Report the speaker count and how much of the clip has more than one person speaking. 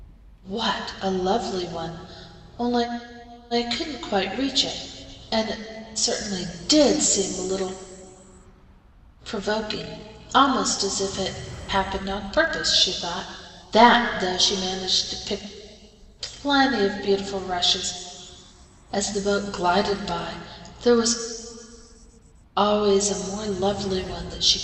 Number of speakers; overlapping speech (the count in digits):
1, no overlap